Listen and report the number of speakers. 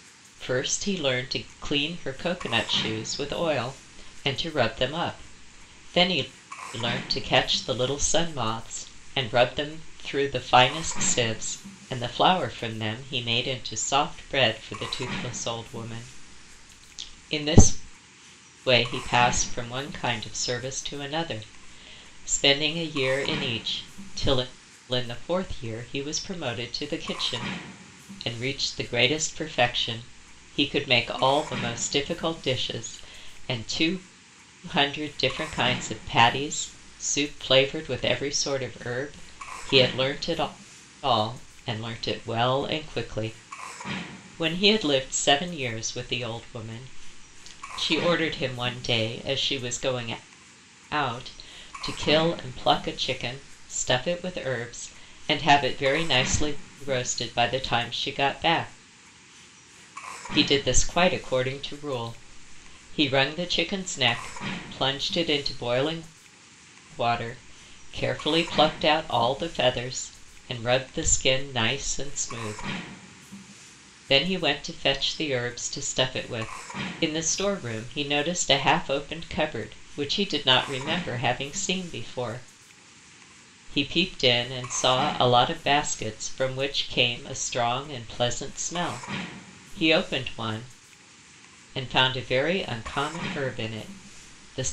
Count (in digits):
1